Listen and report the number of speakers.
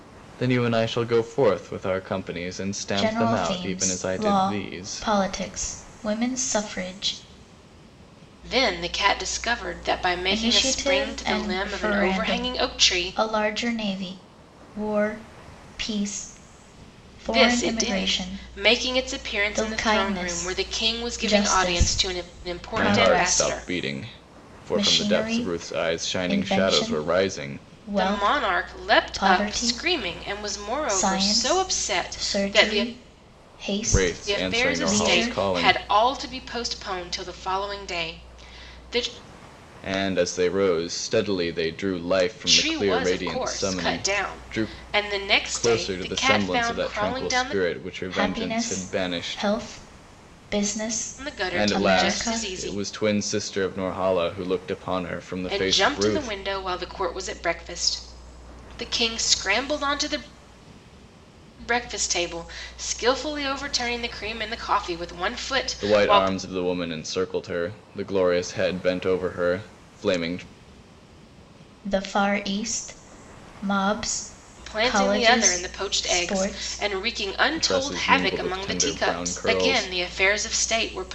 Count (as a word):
three